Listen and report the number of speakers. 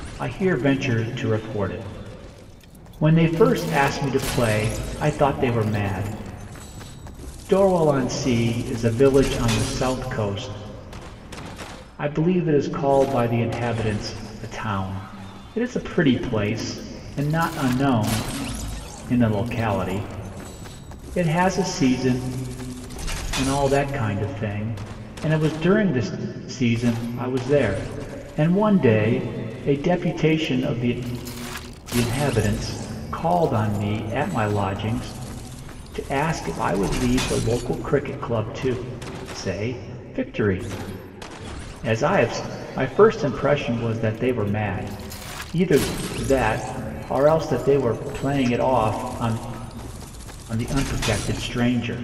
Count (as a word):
one